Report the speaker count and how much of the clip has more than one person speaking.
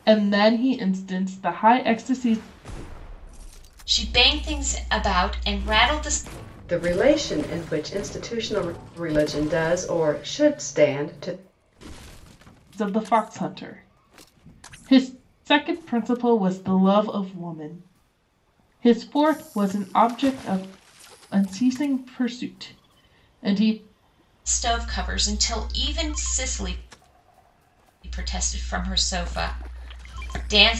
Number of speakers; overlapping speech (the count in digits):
3, no overlap